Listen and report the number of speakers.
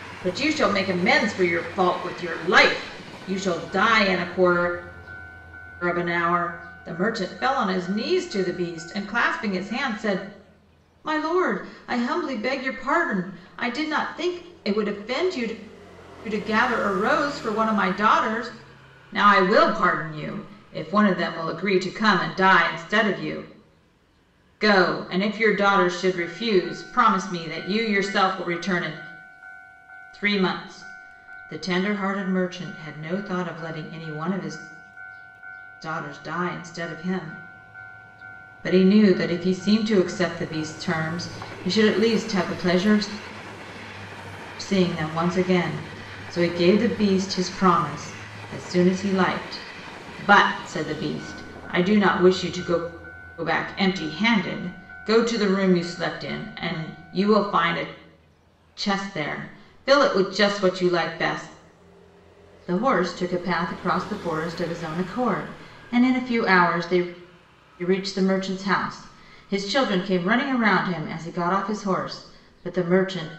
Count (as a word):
one